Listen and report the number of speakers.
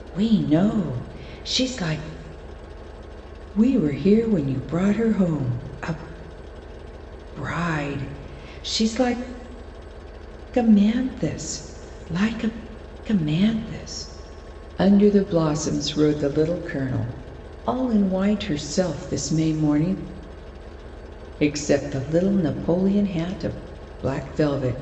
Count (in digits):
1